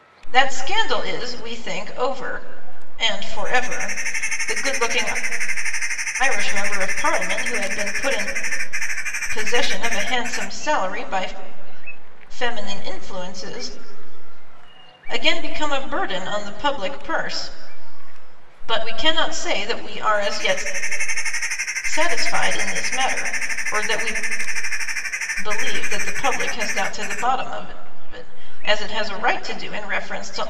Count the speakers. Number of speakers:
1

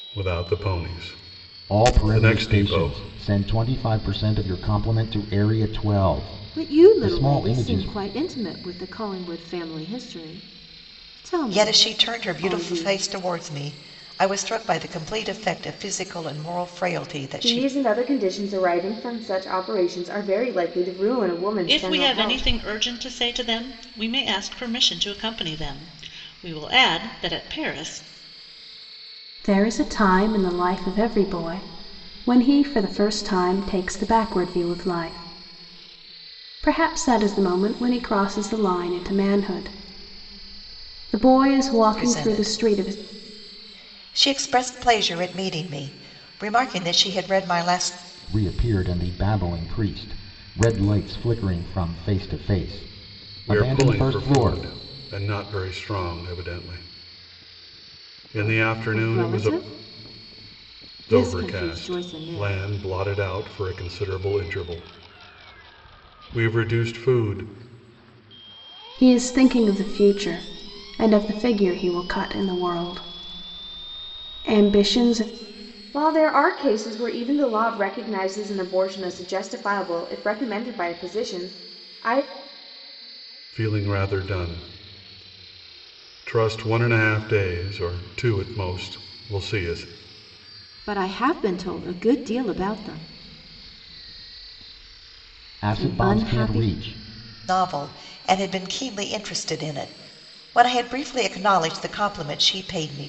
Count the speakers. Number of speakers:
7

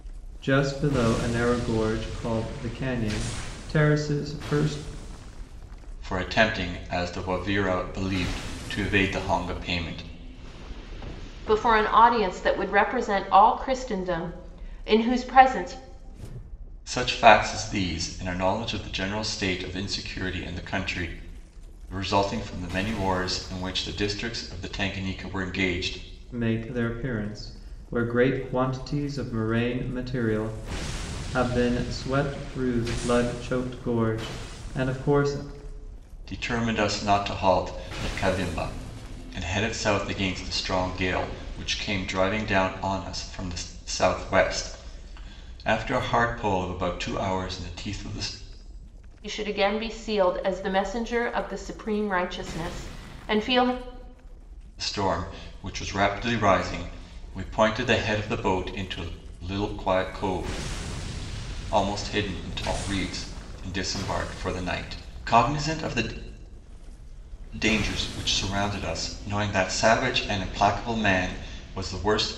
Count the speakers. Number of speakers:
3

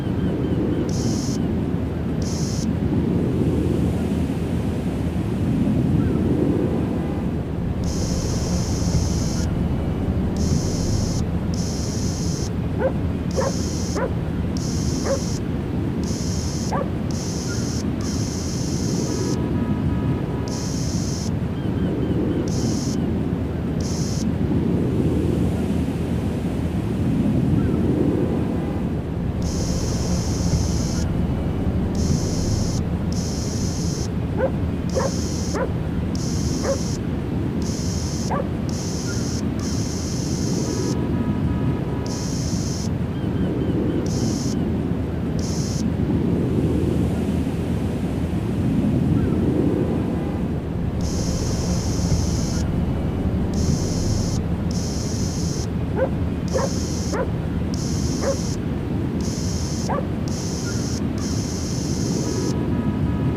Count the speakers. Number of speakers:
0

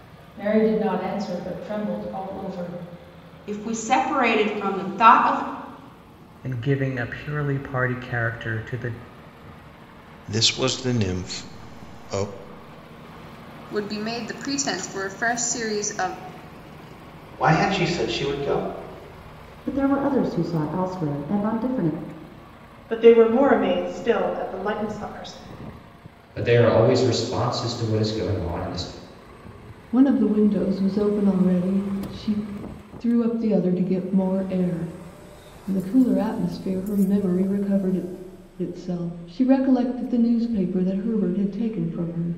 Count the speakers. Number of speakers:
10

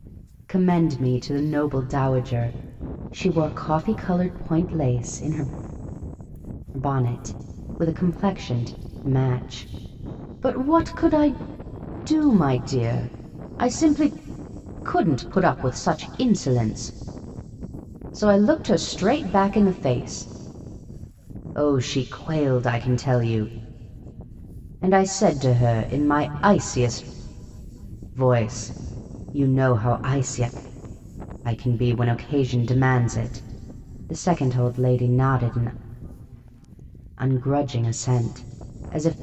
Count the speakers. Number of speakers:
1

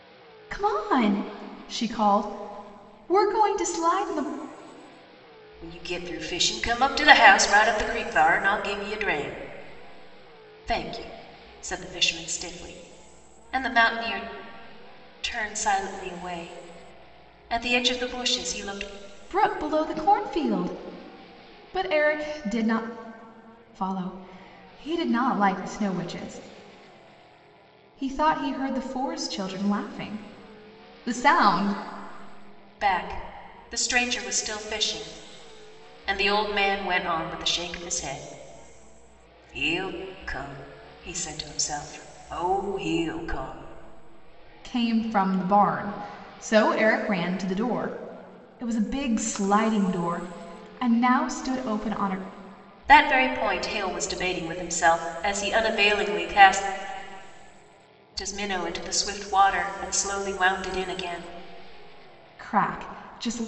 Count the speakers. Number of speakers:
2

